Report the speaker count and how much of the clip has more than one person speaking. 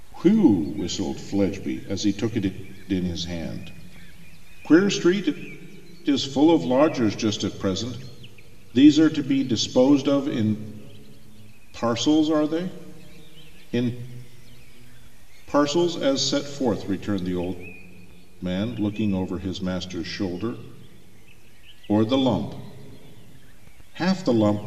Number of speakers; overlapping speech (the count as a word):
one, no overlap